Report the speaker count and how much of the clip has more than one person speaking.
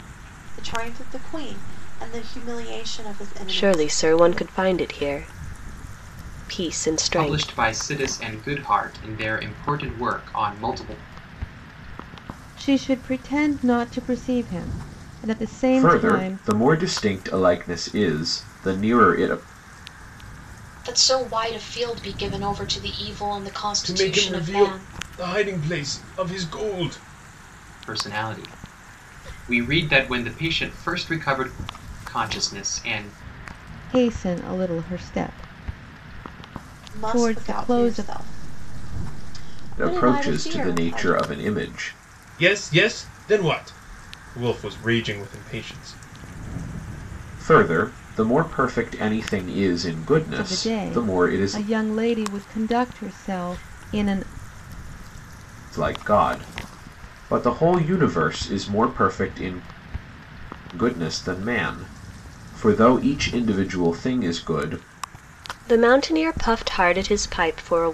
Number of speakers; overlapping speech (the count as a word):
seven, about 11%